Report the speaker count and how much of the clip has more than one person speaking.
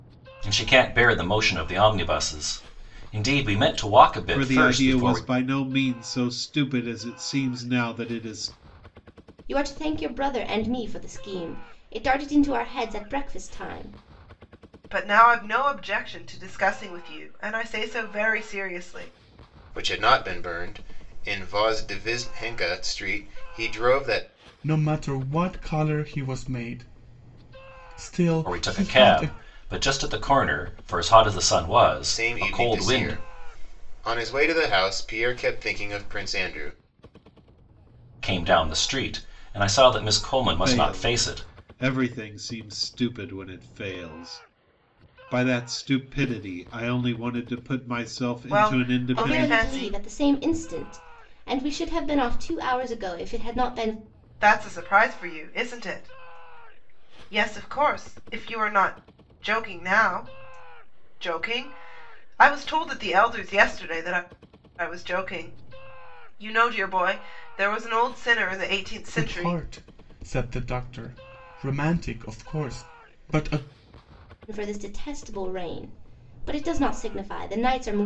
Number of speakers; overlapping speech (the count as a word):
six, about 8%